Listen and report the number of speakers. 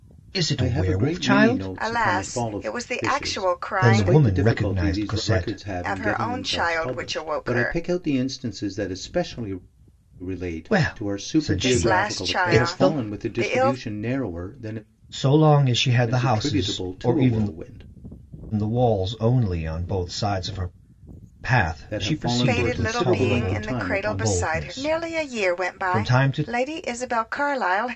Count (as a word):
three